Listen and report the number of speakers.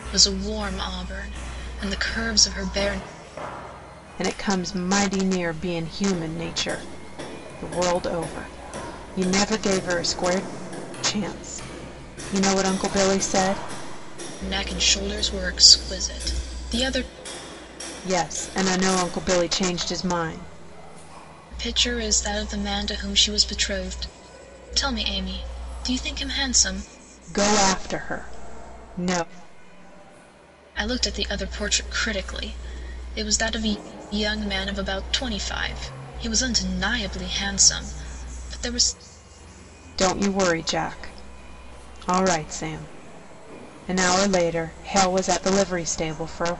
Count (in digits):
2